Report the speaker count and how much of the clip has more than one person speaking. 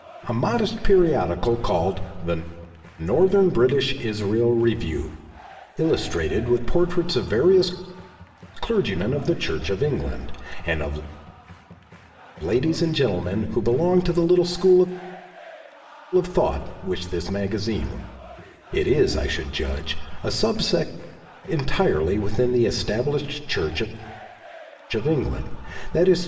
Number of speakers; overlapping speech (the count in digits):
1, no overlap